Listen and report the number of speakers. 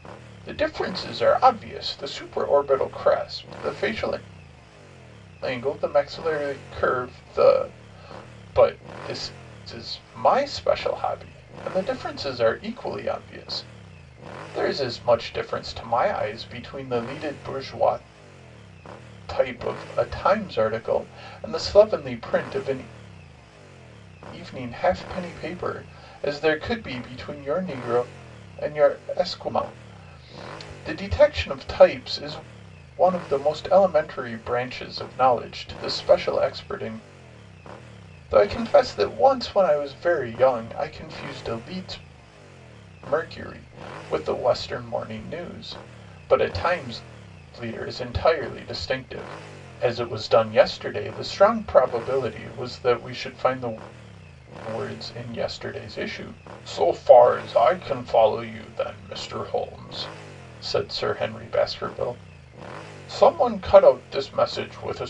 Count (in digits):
1